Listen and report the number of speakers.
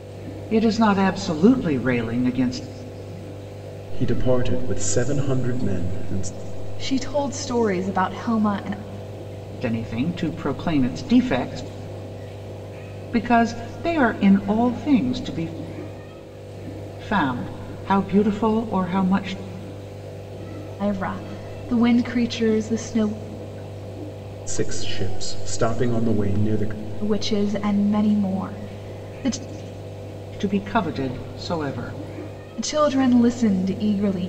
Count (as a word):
three